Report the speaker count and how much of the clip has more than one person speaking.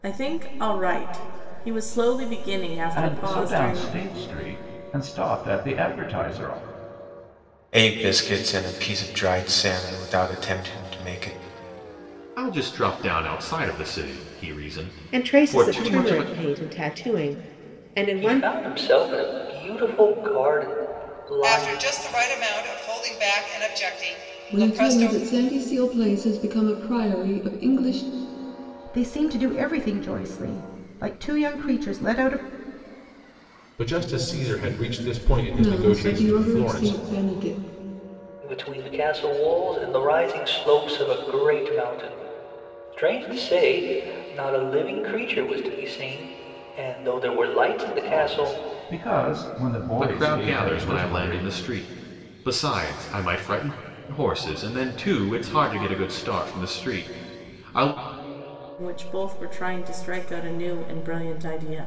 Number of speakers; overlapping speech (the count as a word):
ten, about 11%